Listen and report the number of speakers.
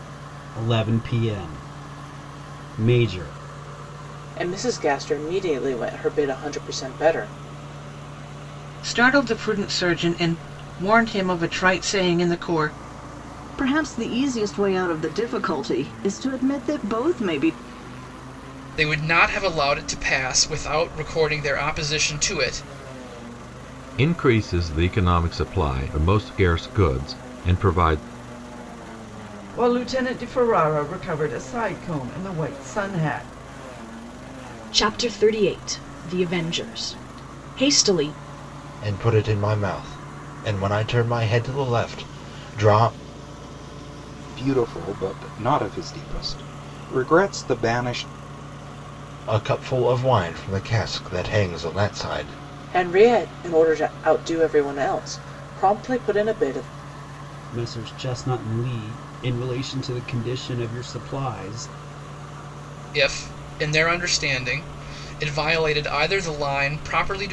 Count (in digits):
10